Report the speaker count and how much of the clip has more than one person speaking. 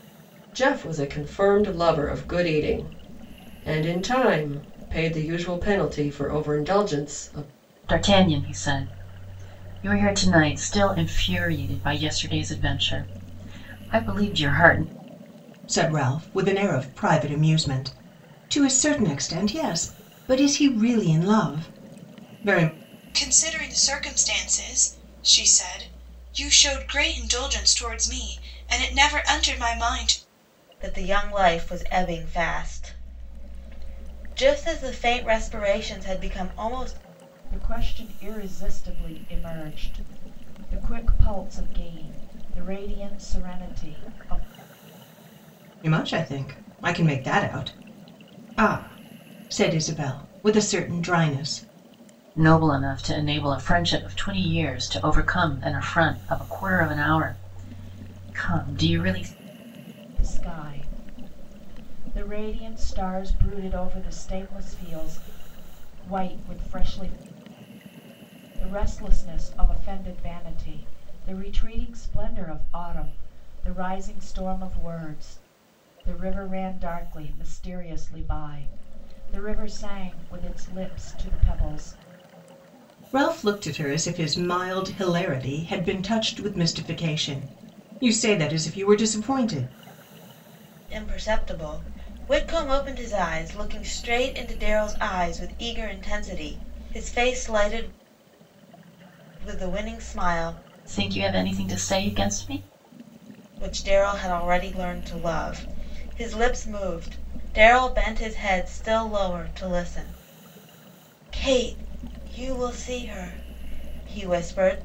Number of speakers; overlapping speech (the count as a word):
six, no overlap